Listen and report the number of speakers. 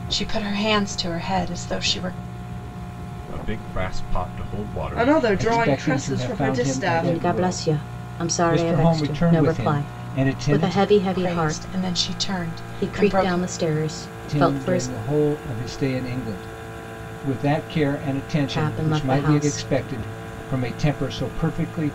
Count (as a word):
five